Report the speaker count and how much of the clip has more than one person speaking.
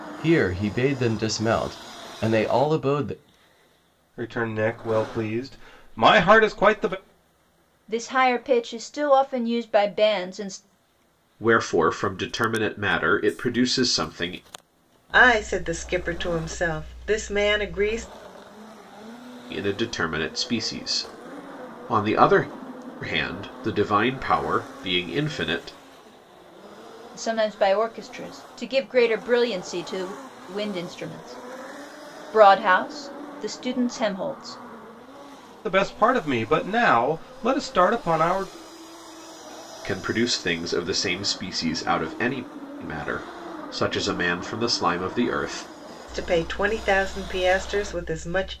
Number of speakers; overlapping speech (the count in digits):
5, no overlap